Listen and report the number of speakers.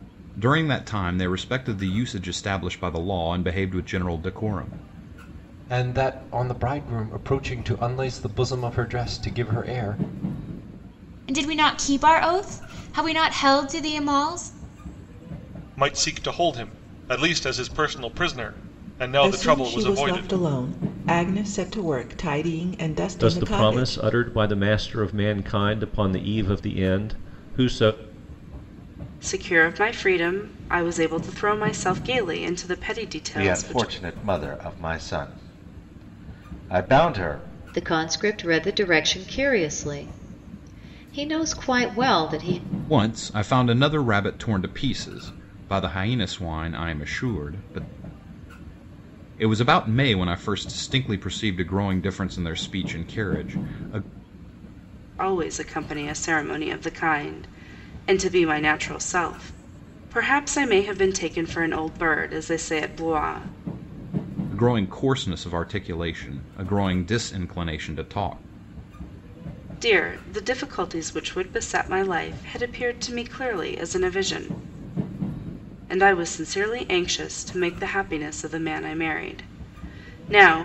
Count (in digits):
9